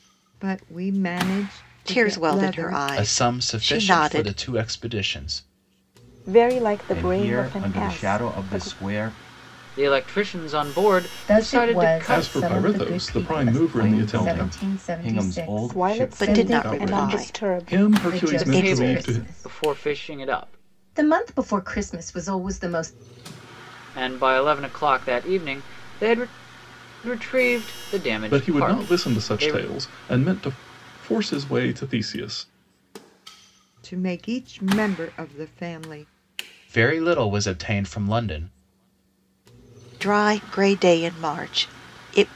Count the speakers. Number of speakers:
eight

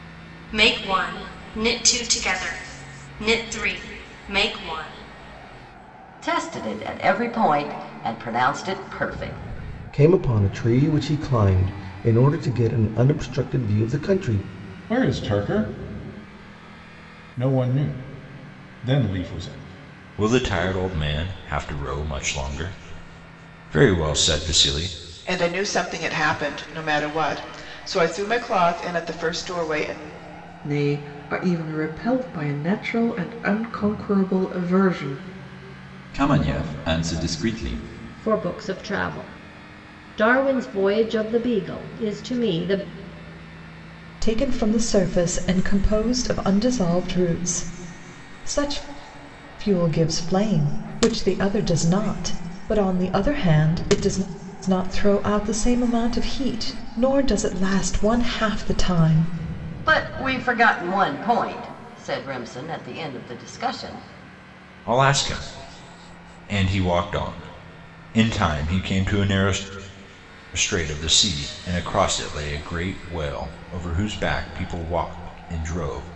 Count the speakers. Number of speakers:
ten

